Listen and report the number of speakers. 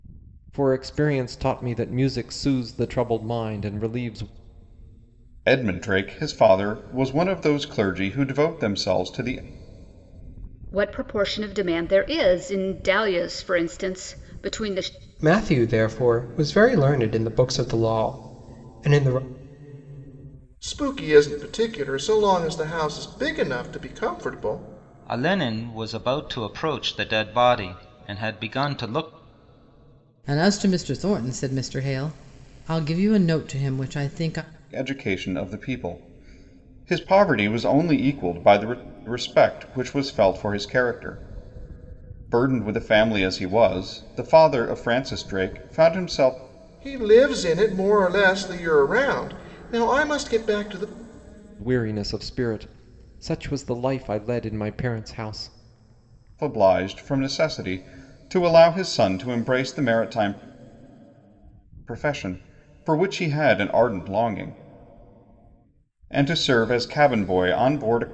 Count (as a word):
seven